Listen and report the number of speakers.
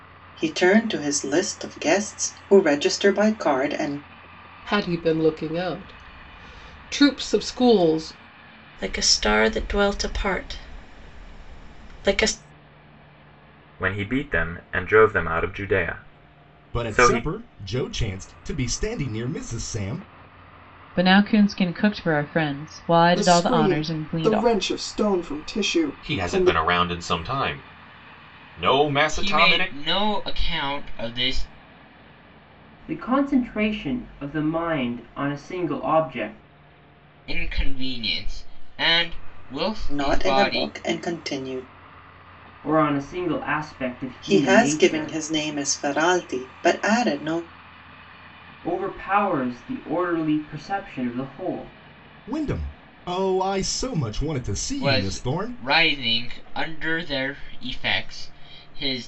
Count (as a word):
ten